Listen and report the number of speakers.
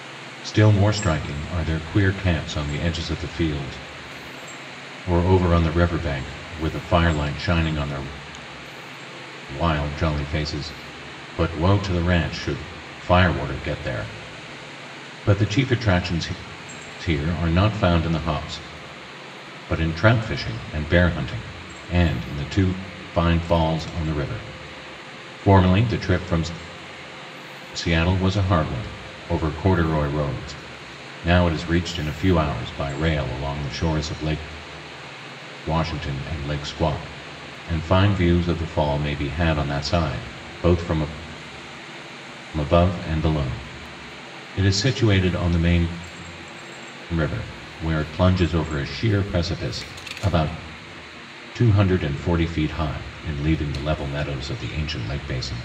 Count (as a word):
one